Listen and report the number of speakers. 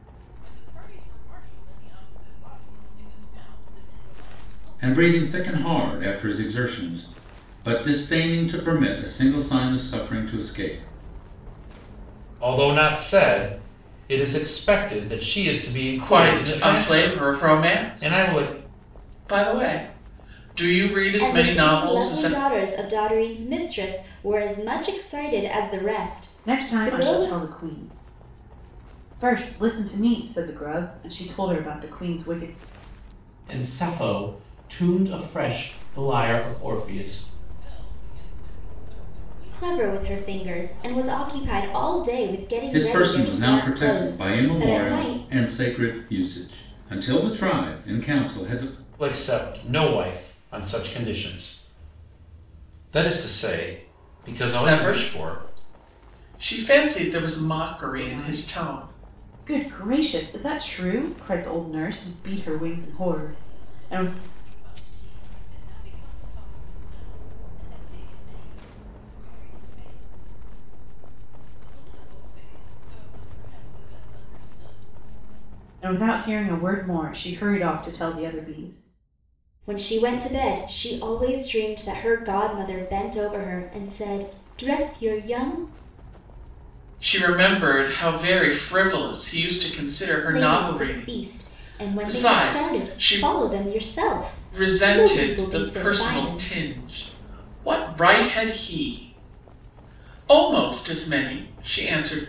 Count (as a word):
seven